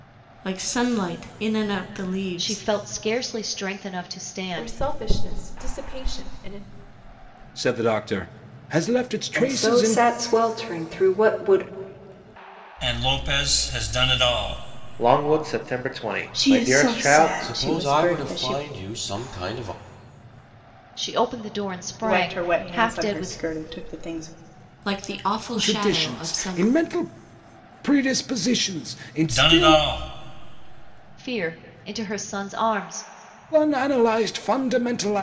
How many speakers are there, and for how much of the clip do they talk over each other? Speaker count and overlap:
9, about 19%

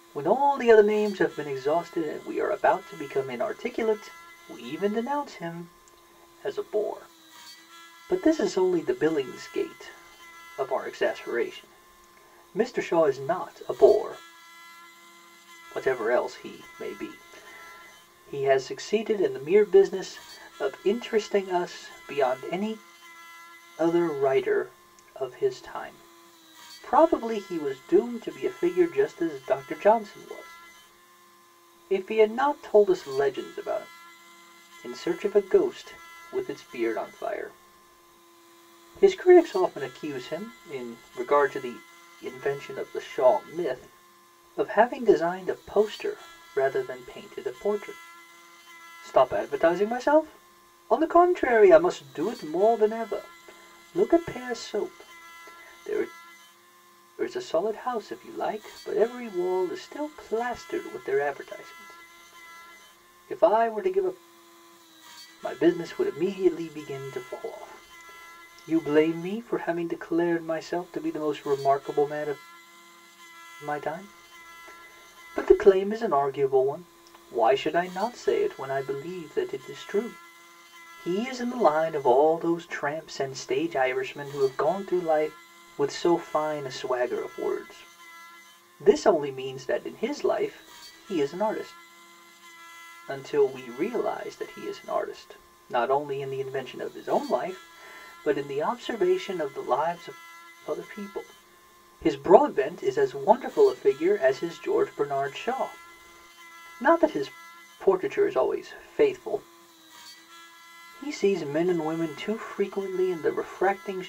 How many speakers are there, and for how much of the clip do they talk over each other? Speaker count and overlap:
1, no overlap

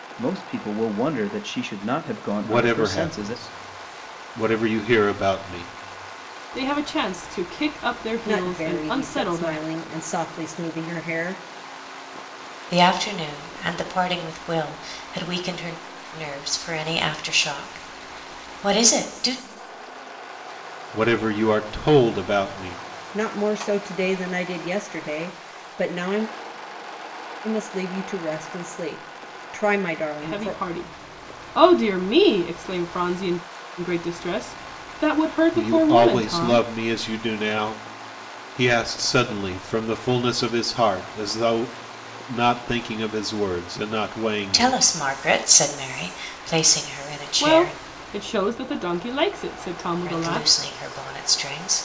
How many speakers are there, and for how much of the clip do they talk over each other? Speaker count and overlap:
5, about 10%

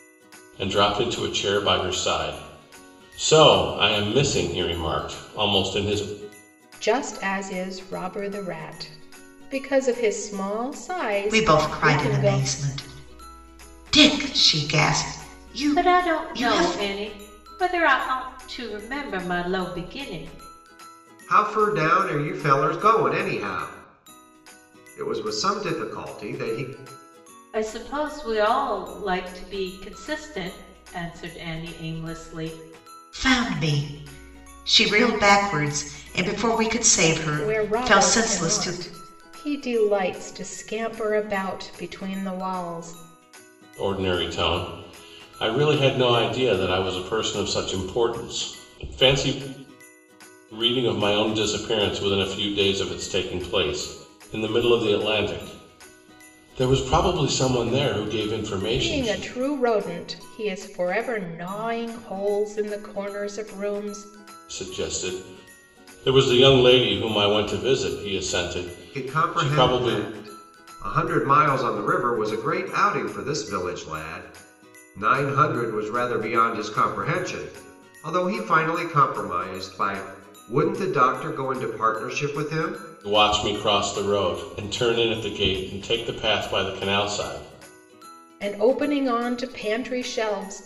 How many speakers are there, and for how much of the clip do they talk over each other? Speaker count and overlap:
5, about 6%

